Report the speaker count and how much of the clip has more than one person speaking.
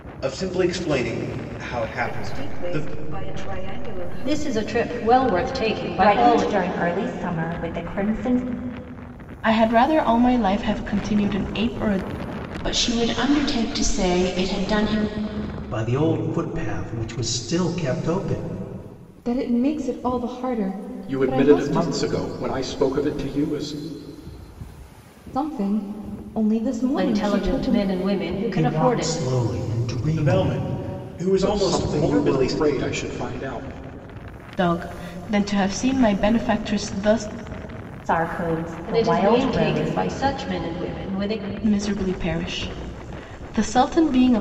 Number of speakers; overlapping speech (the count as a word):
nine, about 16%